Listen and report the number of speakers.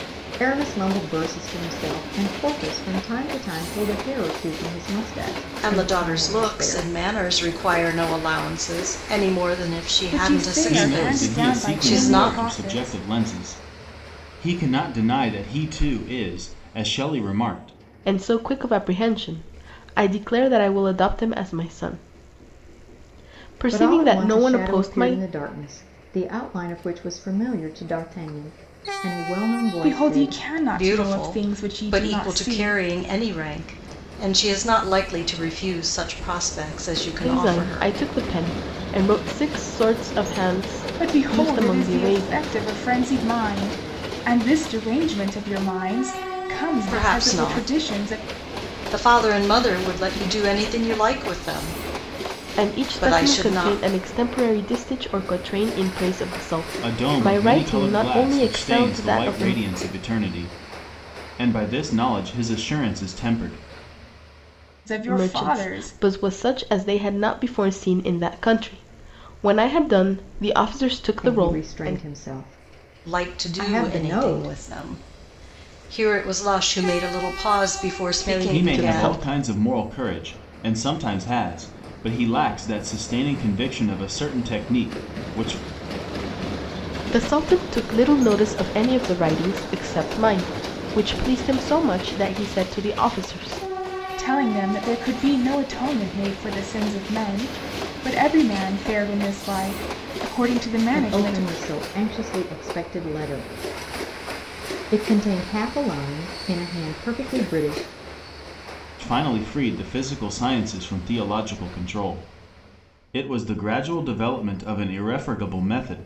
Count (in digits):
5